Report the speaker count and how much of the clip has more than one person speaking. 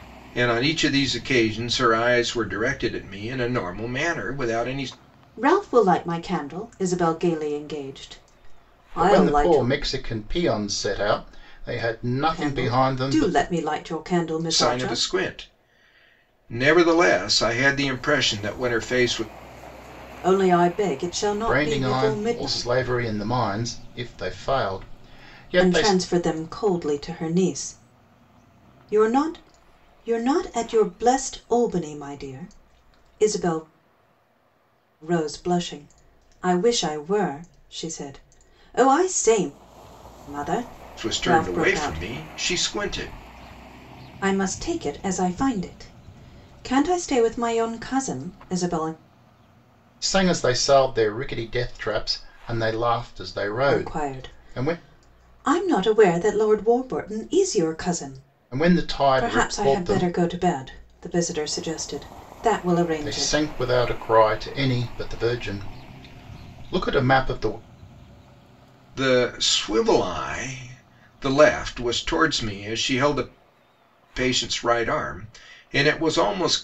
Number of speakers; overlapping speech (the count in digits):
3, about 11%